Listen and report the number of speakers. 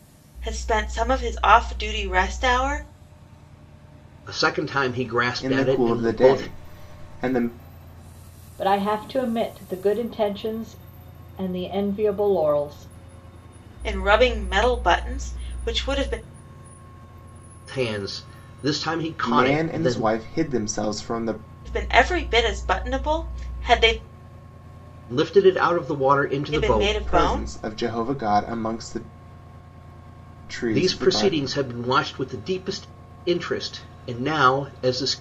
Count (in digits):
4